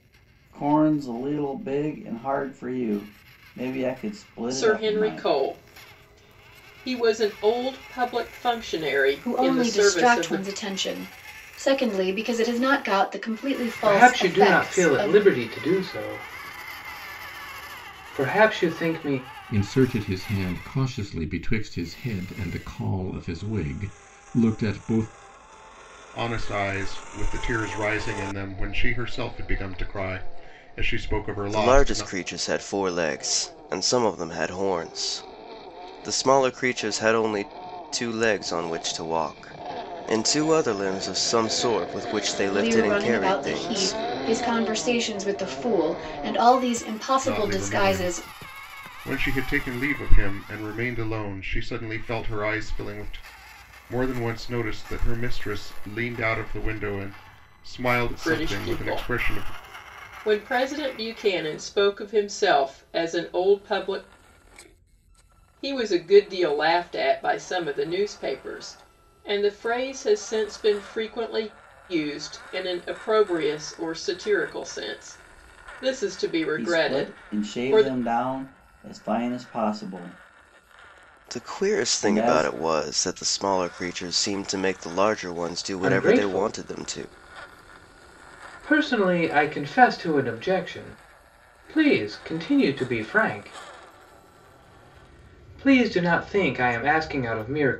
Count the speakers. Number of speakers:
7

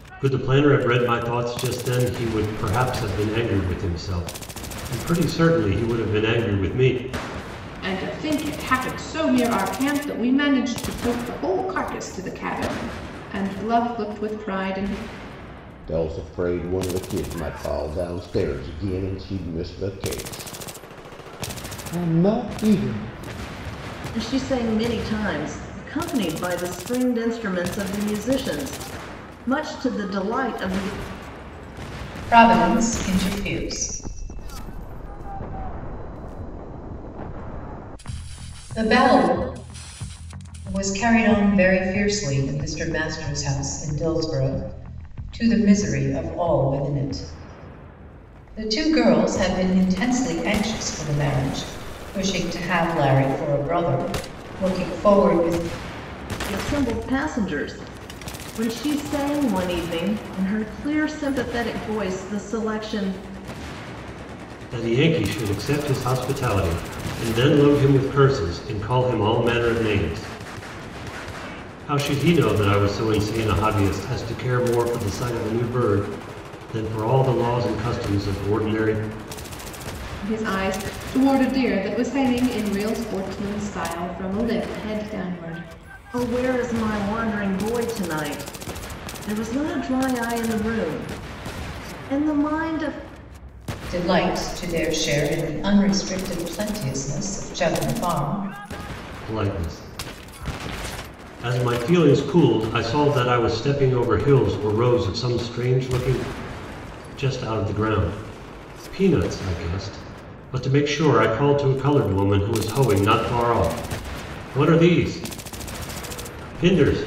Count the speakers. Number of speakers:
5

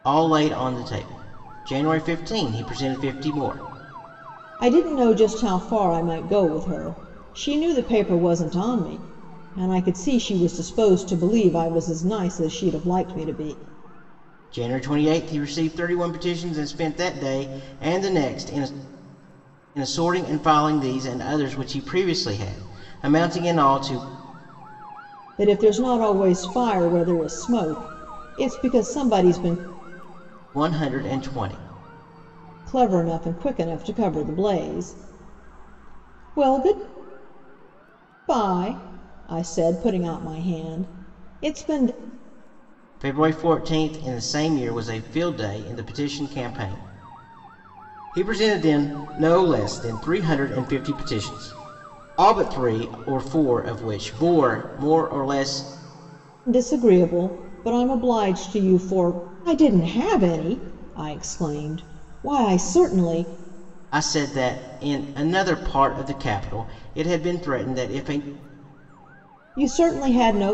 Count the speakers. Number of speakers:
2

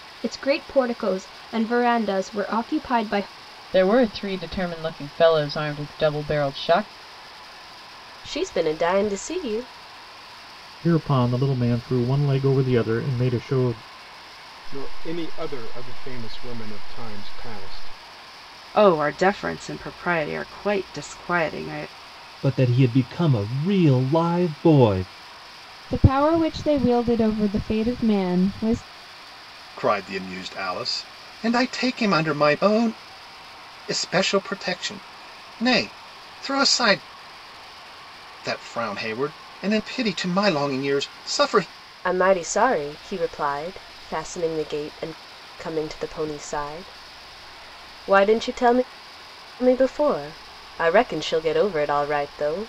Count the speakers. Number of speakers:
9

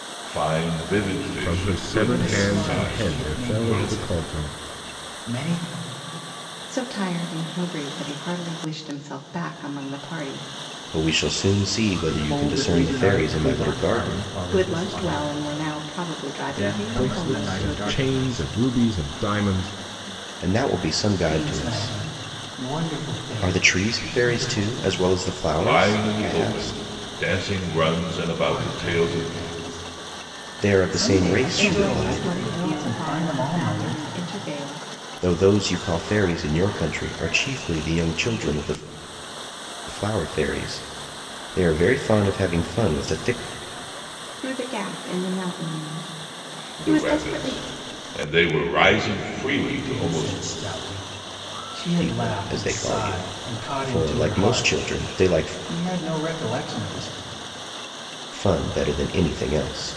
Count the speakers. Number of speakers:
6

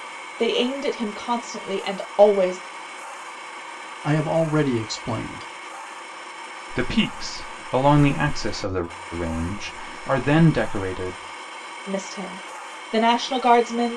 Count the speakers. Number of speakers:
3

